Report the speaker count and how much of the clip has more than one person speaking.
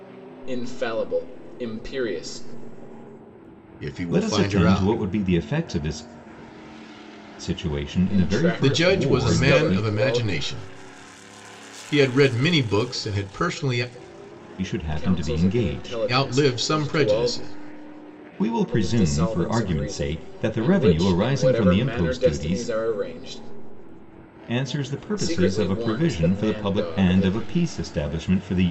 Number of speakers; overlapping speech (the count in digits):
3, about 41%